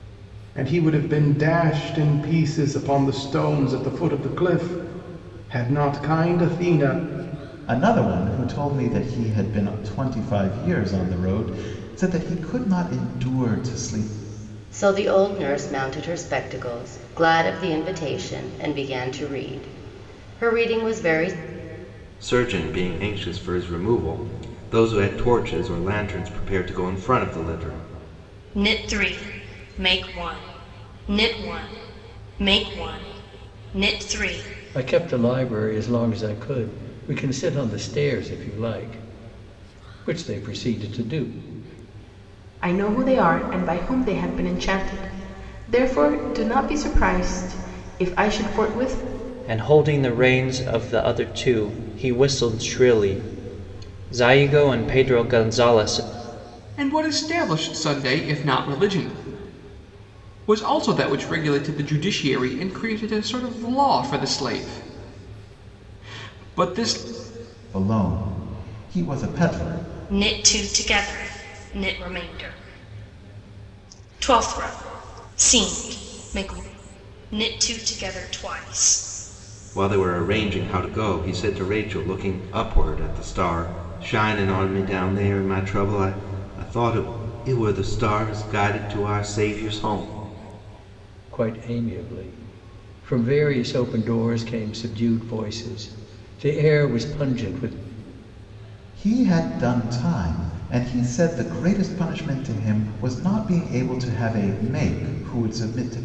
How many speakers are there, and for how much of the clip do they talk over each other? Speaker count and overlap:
nine, no overlap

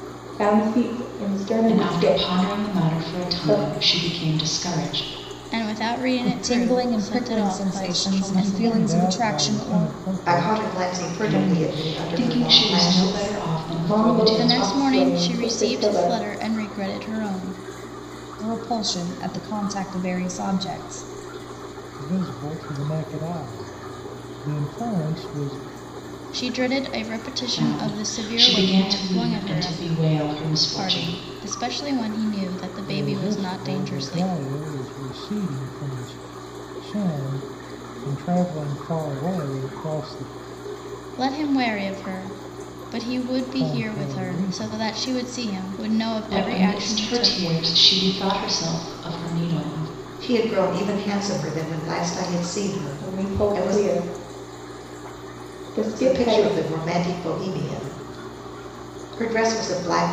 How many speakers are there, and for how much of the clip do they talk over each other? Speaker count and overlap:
six, about 33%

